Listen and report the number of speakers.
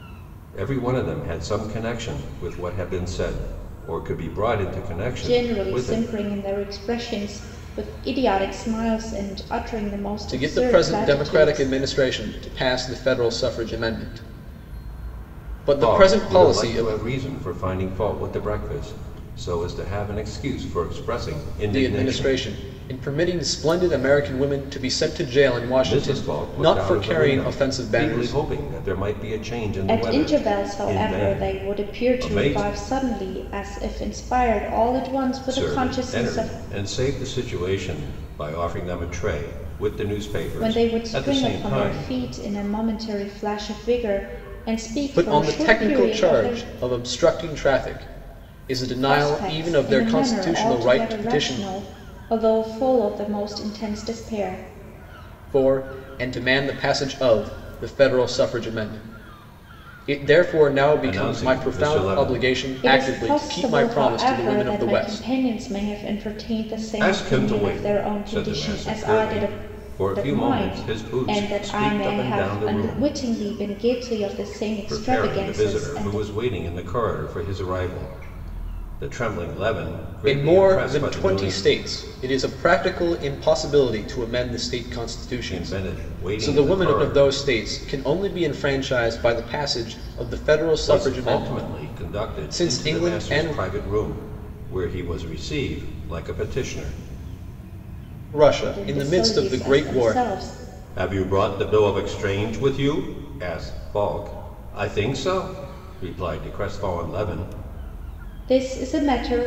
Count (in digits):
3